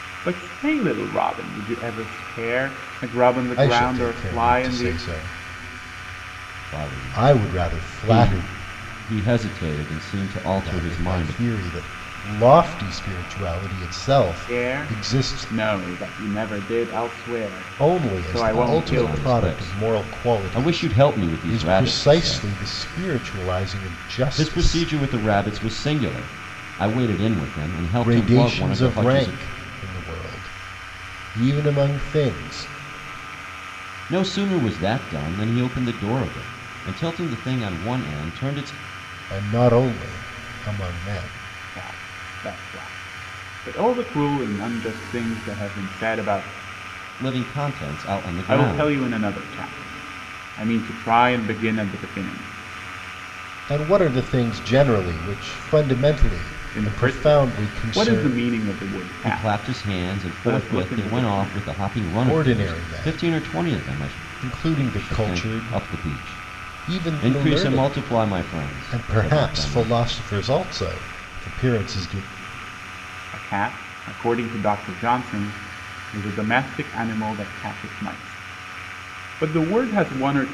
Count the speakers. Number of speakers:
3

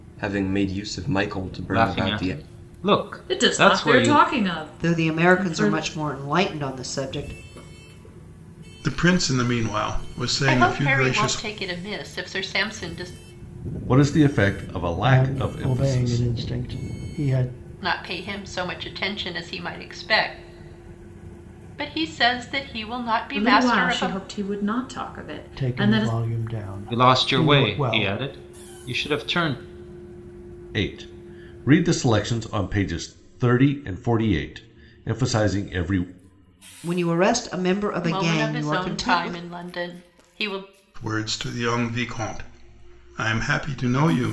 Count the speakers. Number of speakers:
8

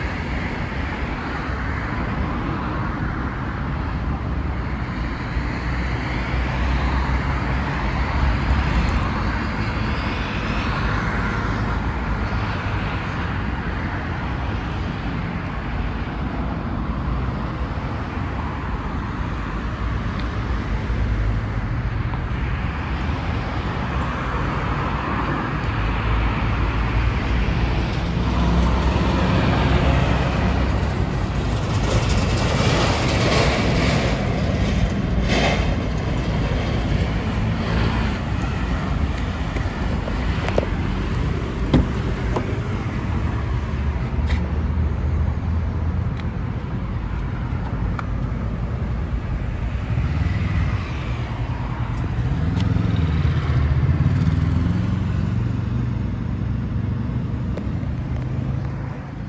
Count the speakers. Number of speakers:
0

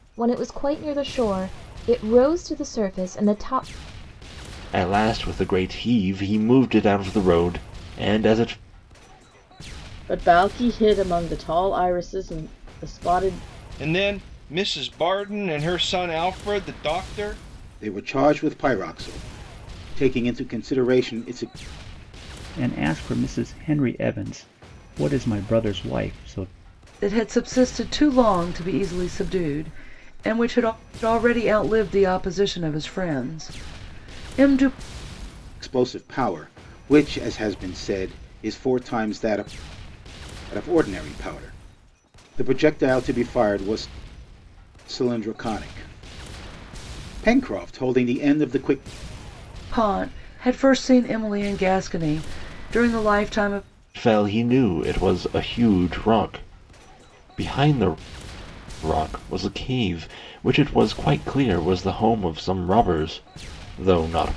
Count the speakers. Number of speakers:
7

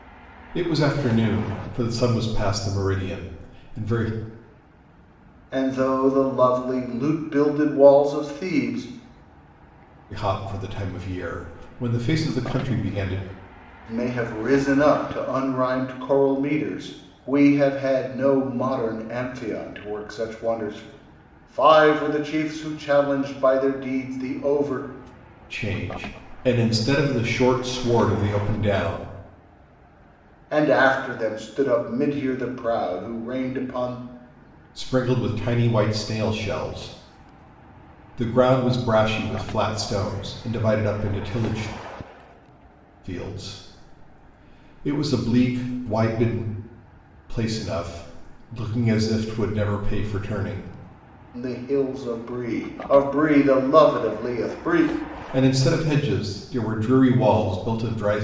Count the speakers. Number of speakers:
2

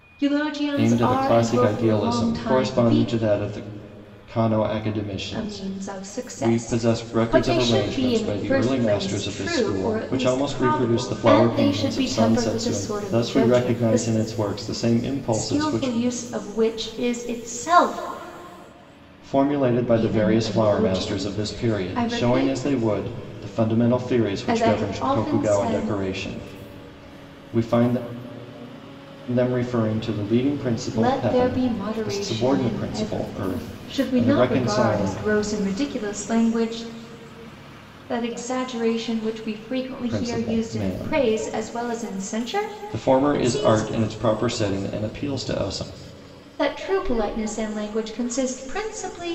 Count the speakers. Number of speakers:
2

